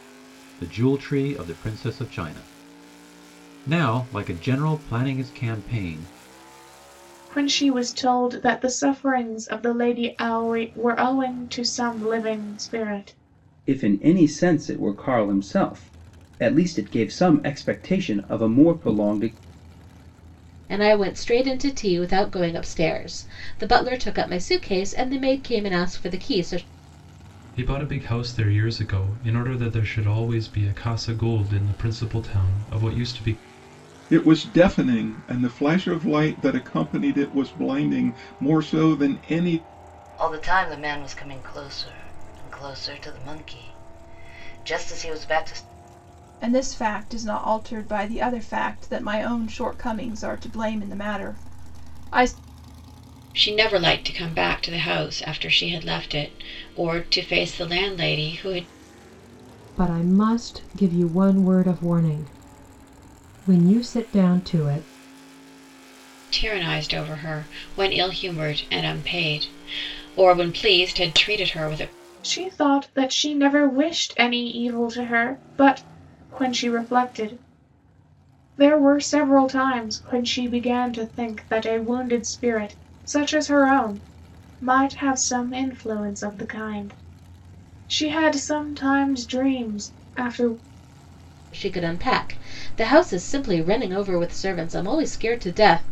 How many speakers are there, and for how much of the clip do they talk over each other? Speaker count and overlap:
10, no overlap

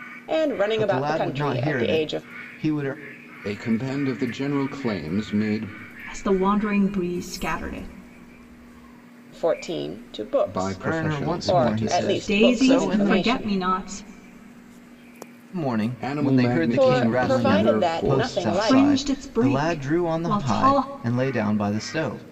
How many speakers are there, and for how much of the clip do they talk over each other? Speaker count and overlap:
4, about 43%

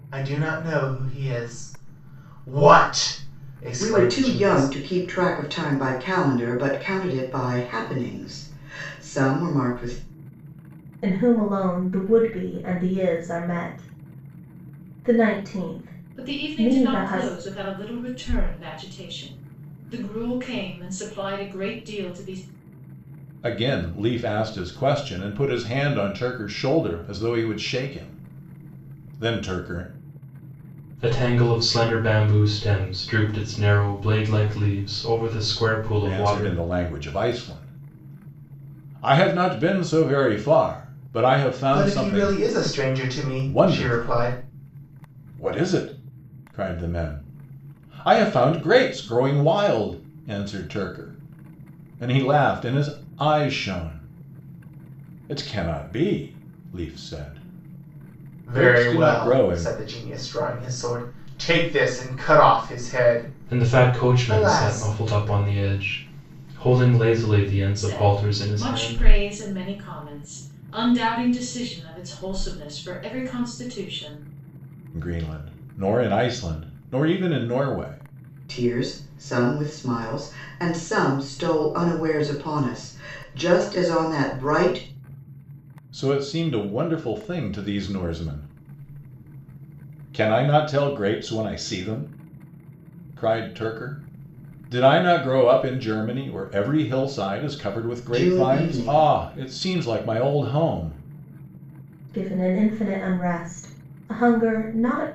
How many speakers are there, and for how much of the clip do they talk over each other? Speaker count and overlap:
6, about 9%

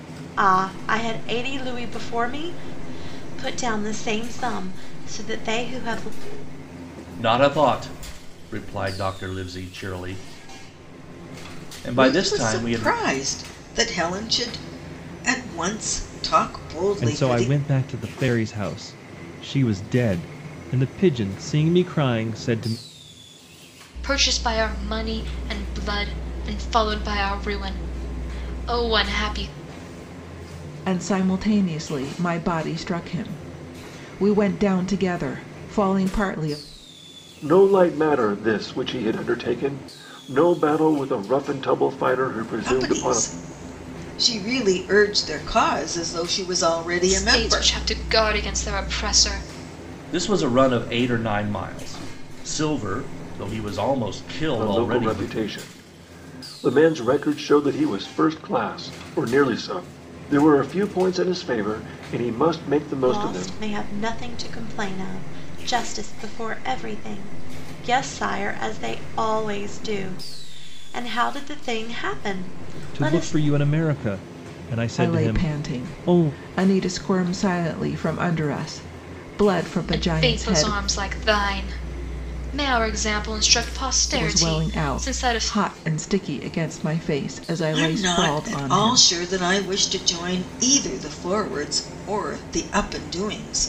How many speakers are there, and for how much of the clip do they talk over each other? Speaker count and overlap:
7, about 10%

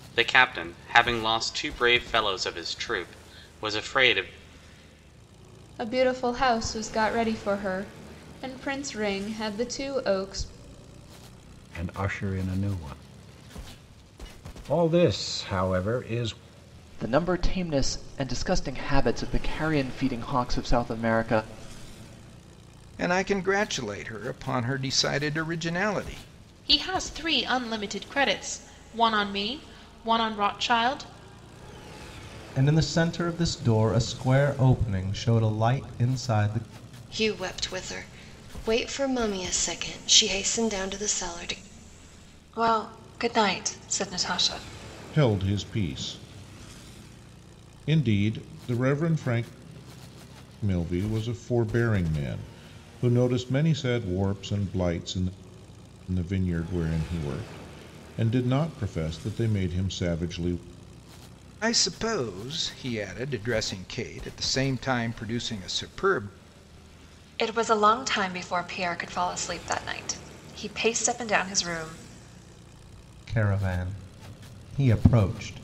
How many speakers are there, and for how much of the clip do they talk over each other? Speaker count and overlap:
10, no overlap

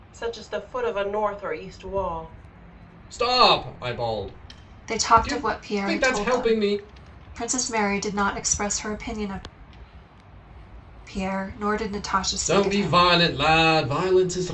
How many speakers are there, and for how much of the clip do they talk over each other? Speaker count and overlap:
3, about 15%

